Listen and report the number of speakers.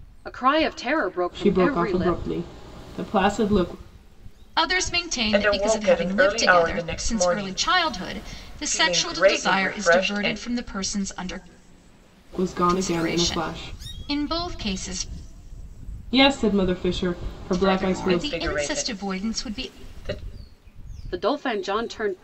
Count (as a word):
four